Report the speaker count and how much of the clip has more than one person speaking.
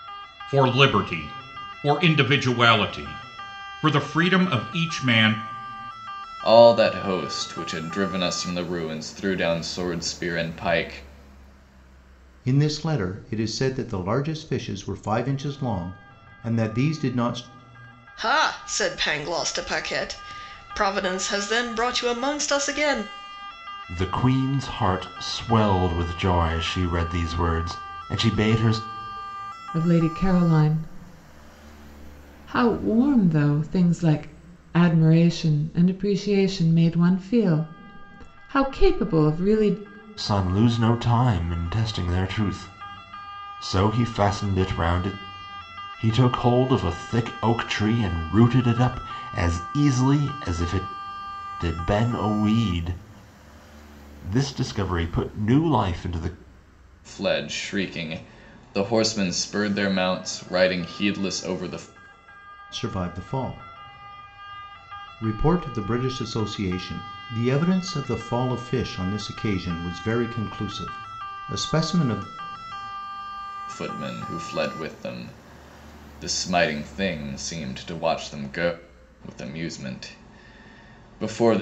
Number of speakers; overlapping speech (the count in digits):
6, no overlap